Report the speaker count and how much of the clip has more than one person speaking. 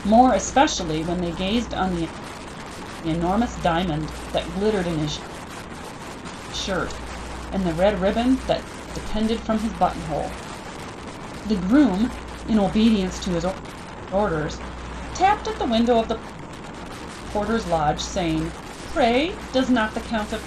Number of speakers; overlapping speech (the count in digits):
1, no overlap